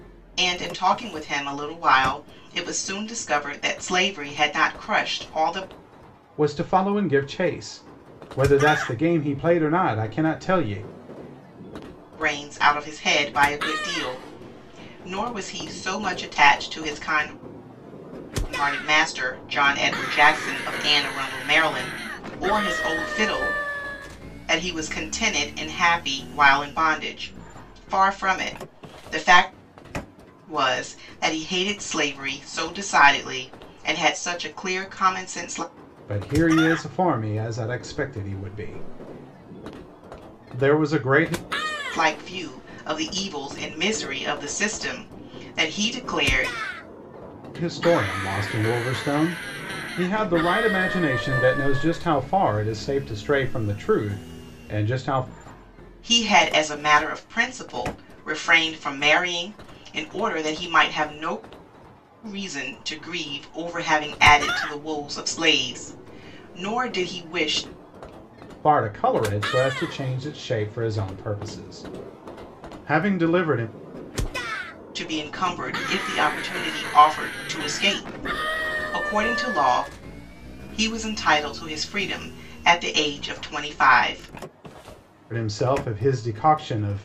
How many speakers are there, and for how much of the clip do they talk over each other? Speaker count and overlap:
2, no overlap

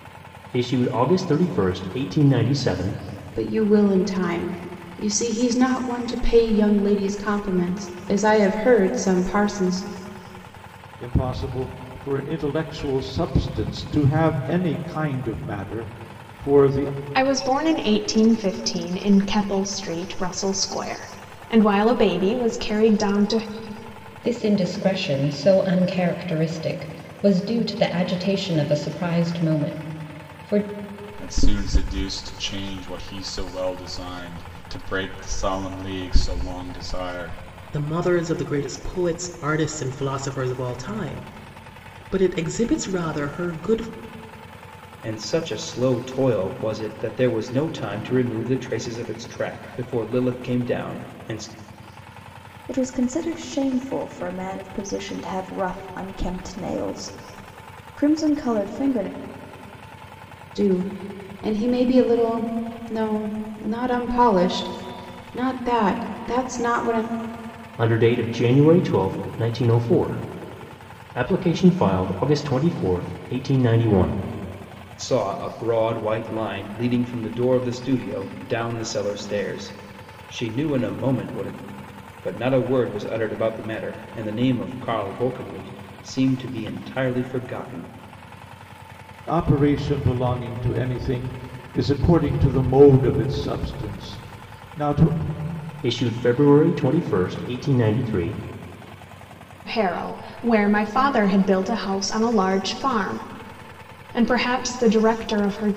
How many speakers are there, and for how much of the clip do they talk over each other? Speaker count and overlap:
9, no overlap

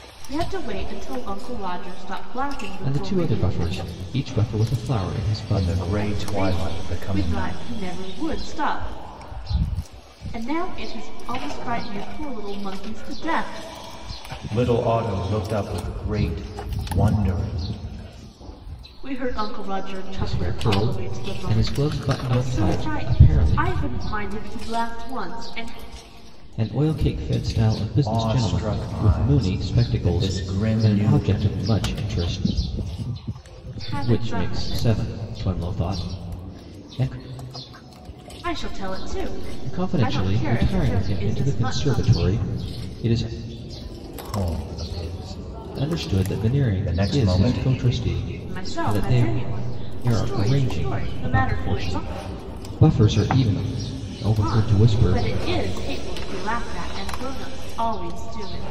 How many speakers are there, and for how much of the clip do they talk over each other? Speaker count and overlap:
3, about 31%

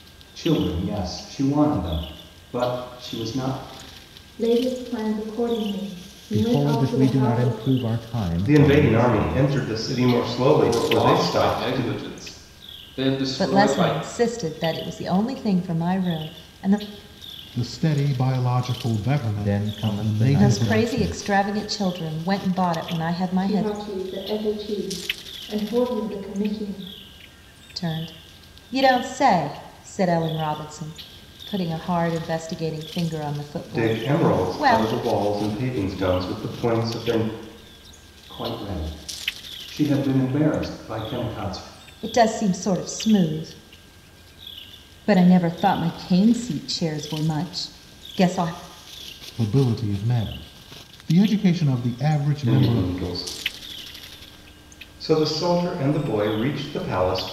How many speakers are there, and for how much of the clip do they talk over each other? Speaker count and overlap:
7, about 15%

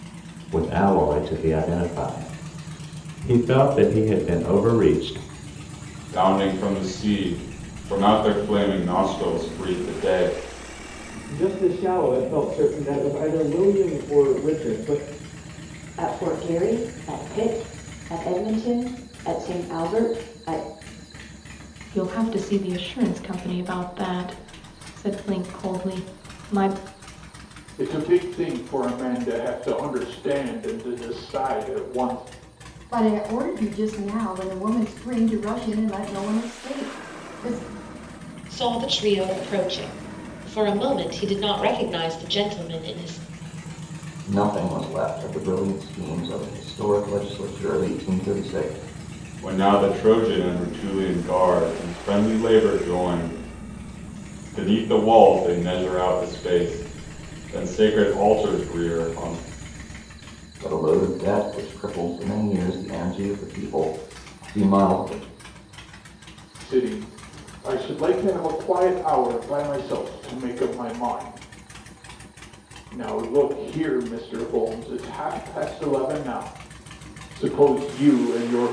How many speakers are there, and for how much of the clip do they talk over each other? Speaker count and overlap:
9, no overlap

